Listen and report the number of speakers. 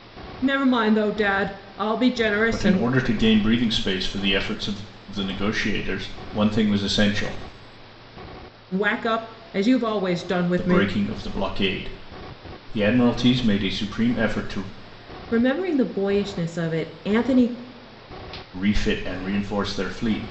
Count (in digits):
2